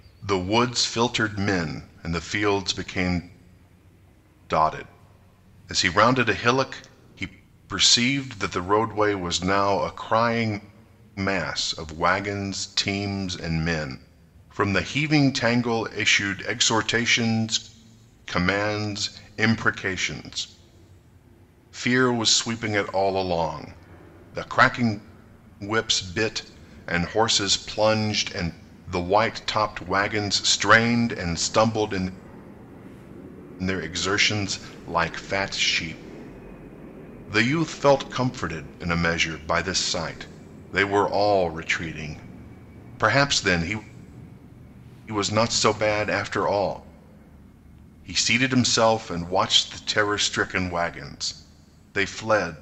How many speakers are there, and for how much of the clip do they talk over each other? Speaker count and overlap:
1, no overlap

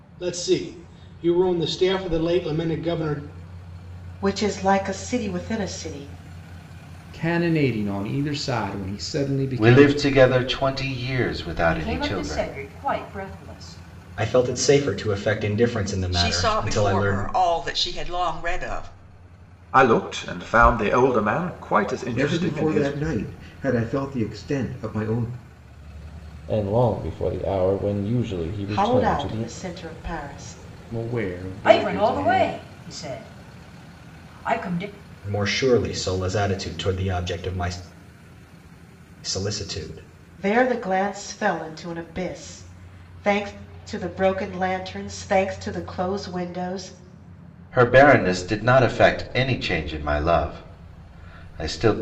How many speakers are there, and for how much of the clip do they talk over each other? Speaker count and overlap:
10, about 10%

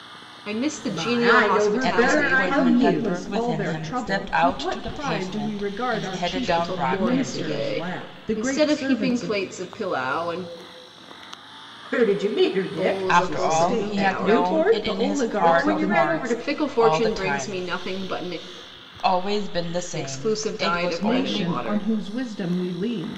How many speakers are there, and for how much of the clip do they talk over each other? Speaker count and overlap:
4, about 66%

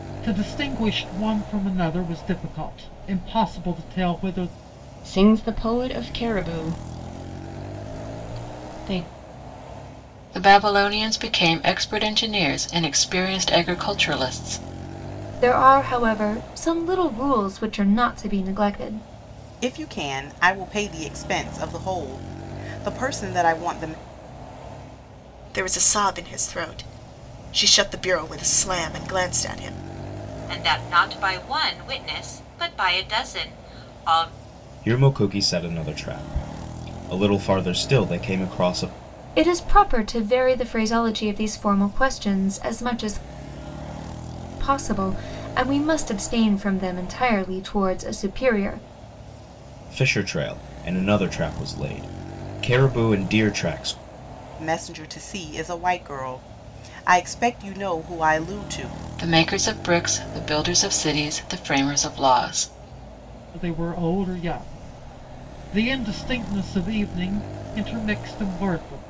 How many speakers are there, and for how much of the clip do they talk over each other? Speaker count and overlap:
8, no overlap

